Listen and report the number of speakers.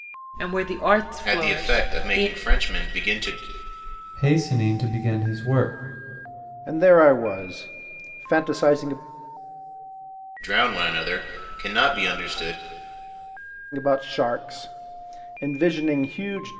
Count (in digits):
4